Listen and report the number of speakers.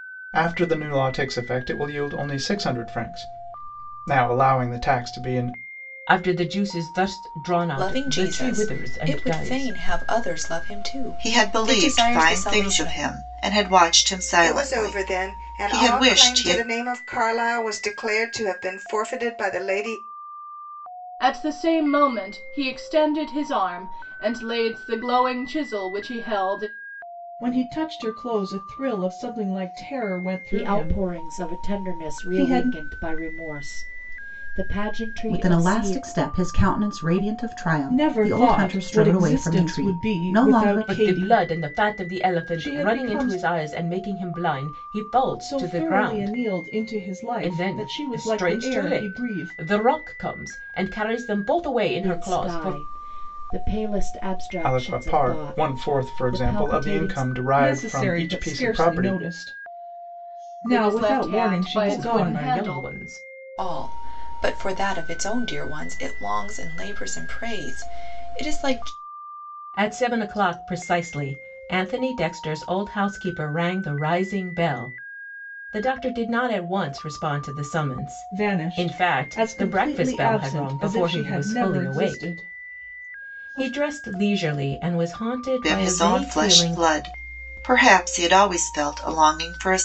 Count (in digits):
9